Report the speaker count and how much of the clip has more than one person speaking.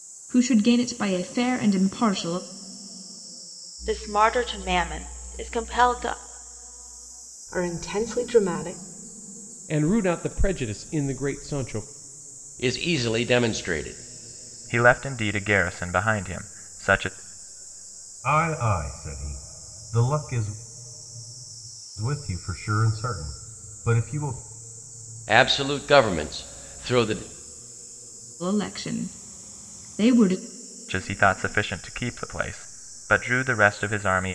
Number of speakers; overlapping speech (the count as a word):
seven, no overlap